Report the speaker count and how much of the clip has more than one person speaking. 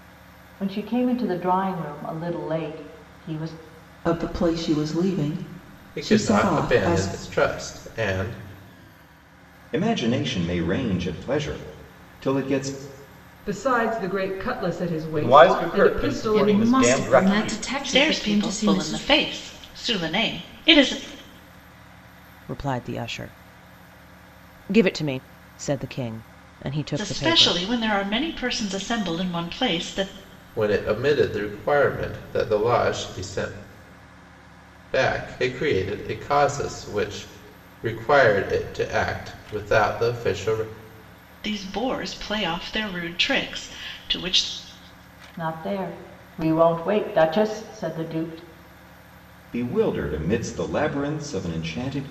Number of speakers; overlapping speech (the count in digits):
9, about 11%